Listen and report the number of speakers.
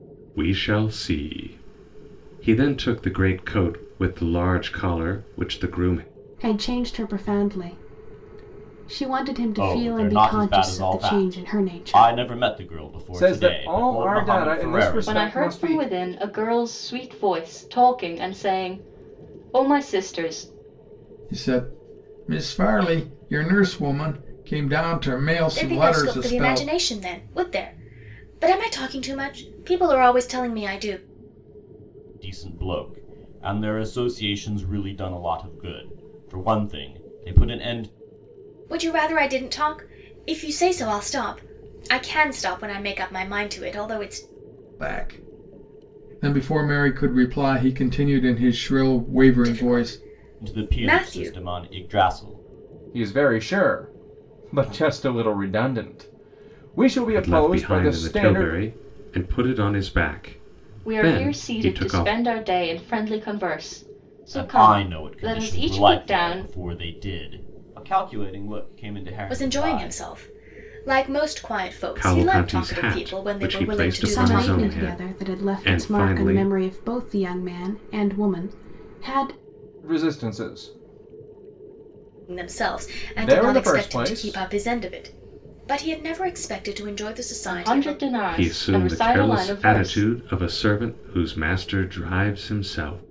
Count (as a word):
seven